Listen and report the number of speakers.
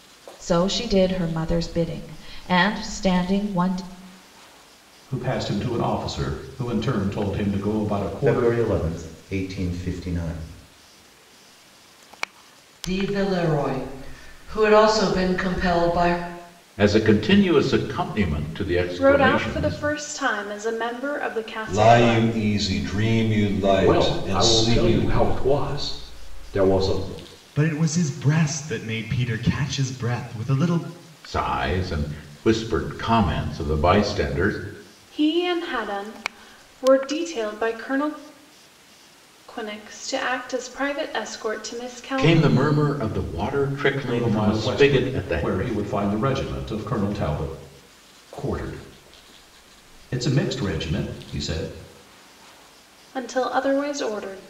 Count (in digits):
9